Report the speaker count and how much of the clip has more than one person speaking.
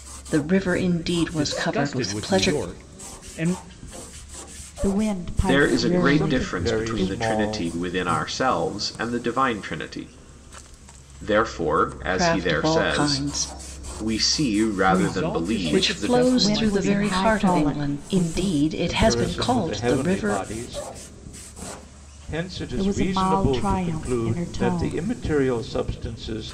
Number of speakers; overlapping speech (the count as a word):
five, about 49%